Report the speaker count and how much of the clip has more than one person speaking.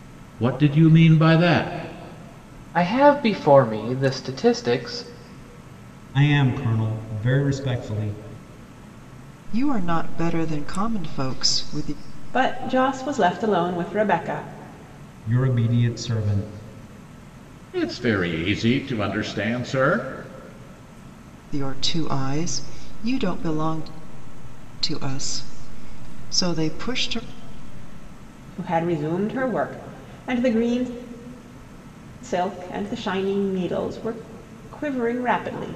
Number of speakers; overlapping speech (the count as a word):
five, no overlap